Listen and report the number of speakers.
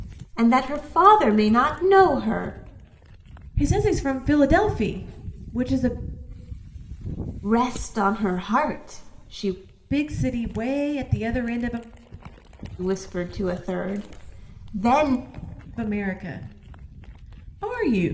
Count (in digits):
2